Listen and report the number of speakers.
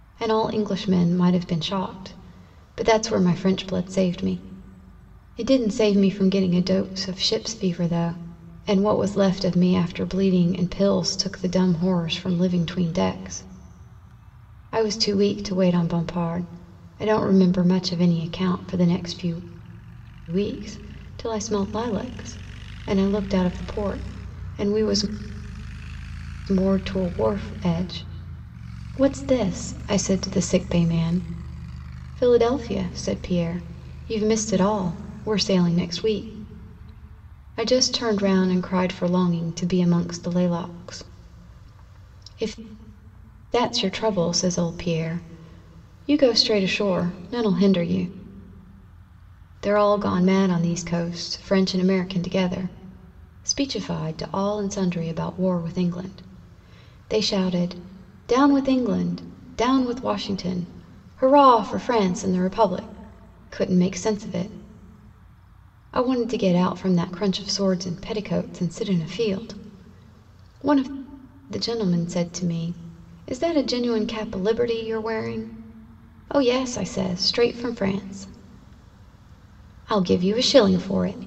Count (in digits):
1